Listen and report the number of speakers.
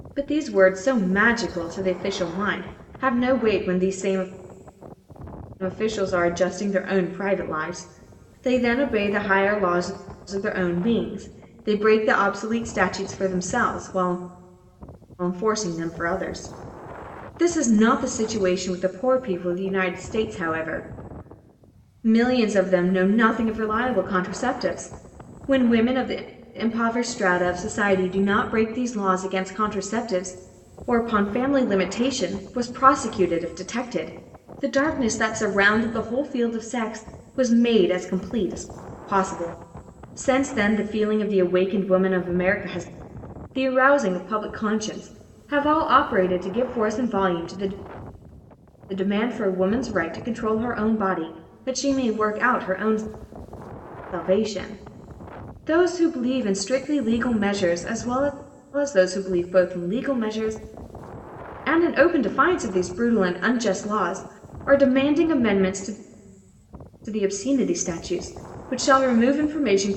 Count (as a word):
one